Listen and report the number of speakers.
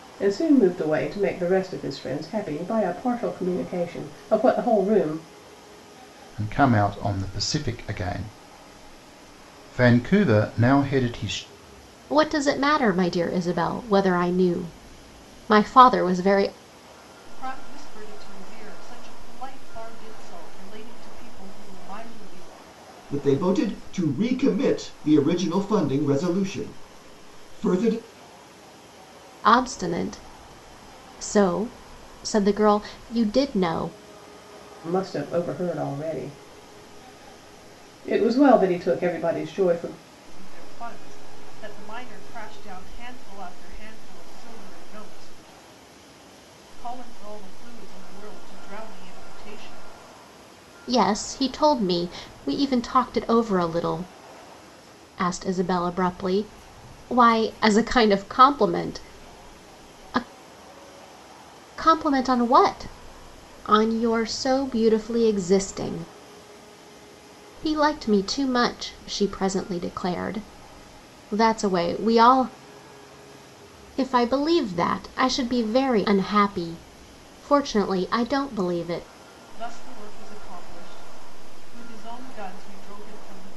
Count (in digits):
5